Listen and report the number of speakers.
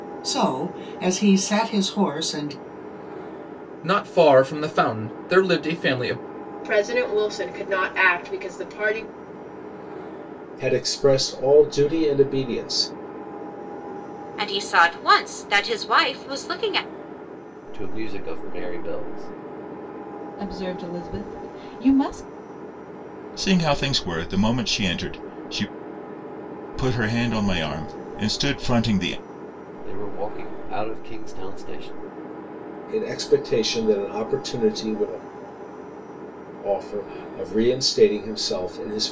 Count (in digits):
8